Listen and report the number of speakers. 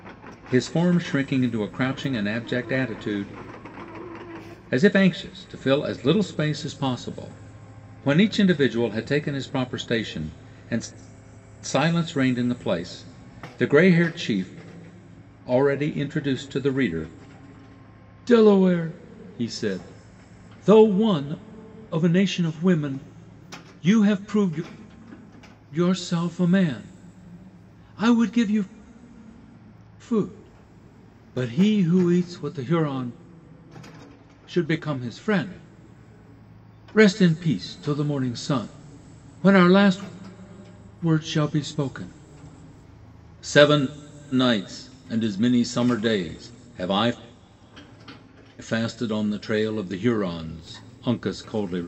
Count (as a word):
one